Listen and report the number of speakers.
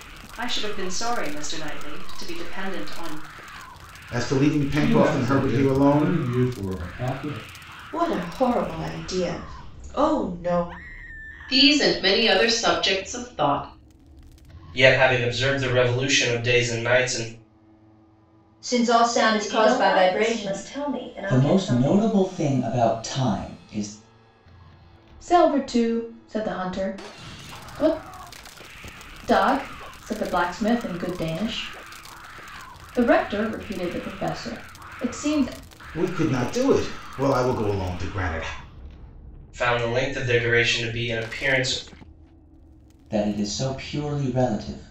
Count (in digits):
10